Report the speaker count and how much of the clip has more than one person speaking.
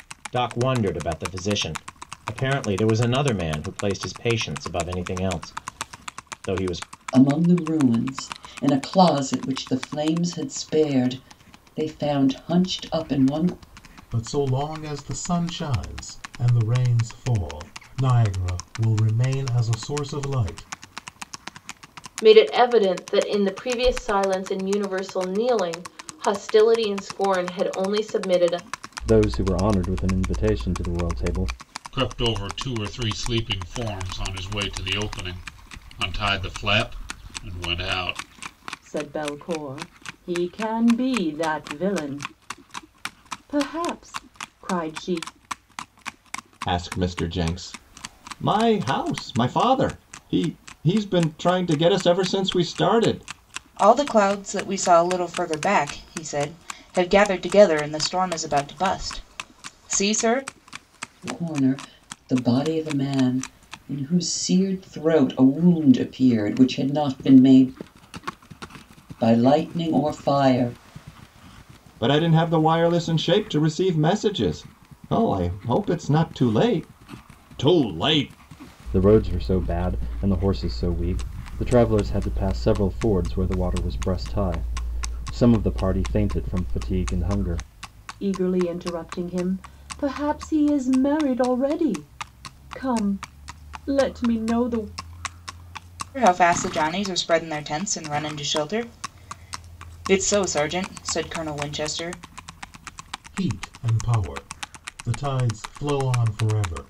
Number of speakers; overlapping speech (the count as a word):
nine, no overlap